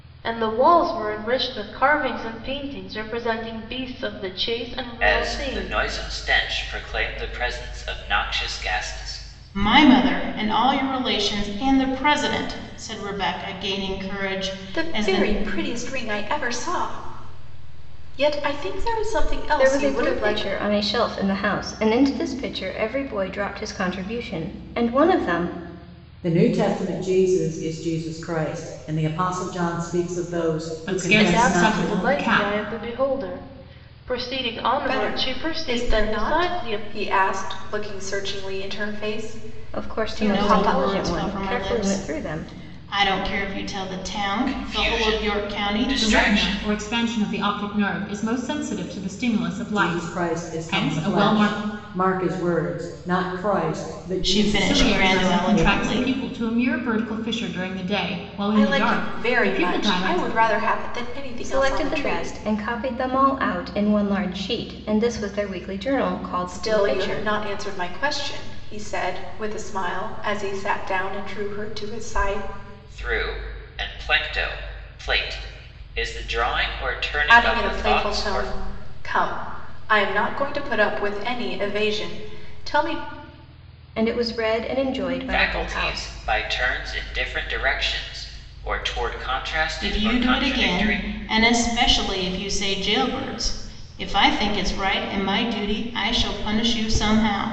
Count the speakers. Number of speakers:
seven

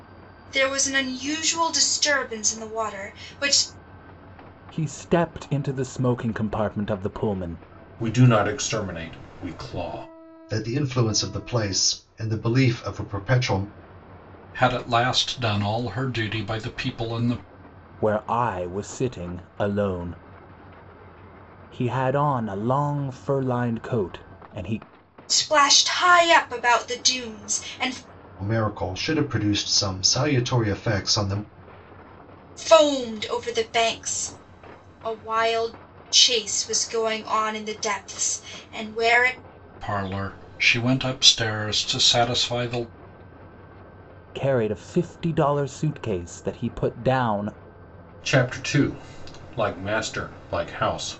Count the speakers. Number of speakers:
five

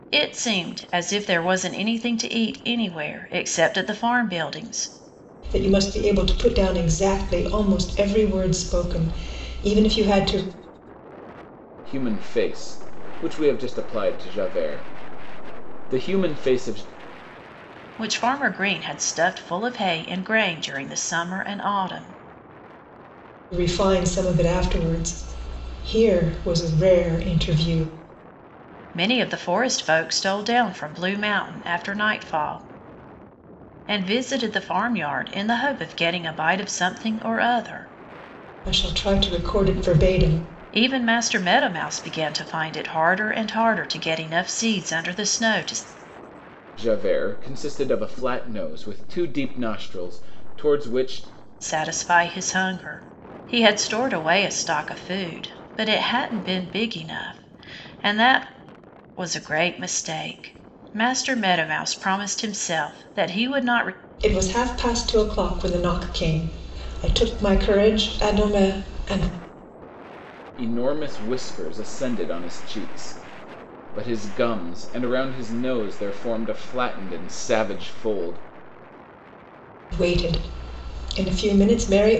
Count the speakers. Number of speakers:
three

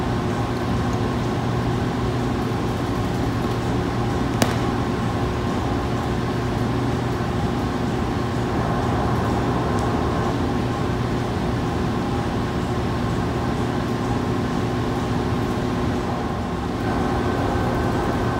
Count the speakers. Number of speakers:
zero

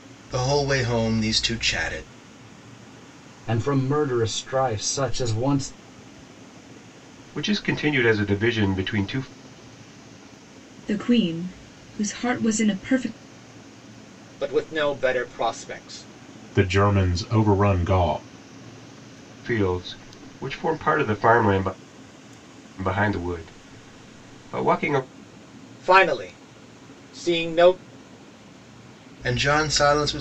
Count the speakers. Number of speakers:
six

